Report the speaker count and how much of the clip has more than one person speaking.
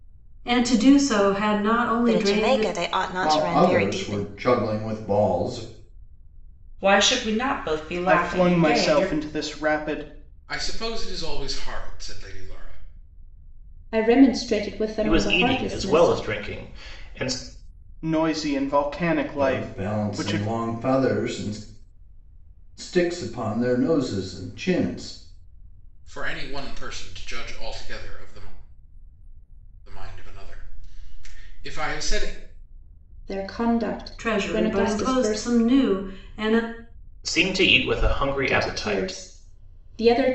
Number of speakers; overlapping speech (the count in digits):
8, about 19%